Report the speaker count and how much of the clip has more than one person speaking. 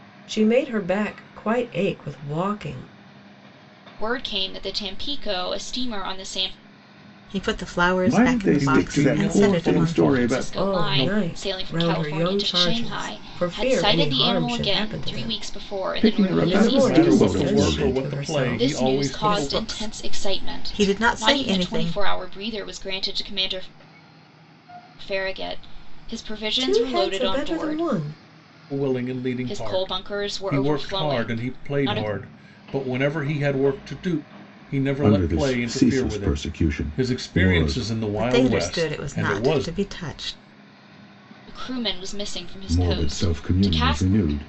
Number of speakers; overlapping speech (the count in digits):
5, about 51%